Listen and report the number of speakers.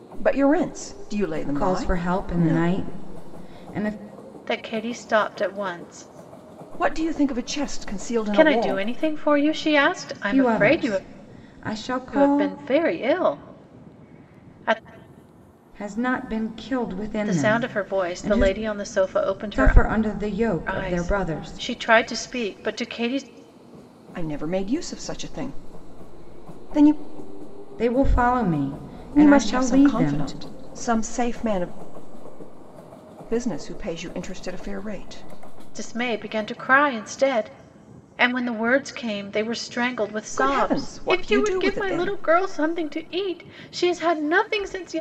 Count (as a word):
three